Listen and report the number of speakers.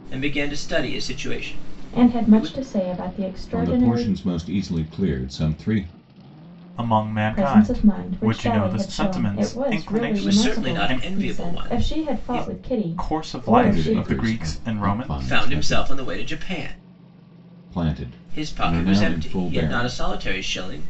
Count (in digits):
4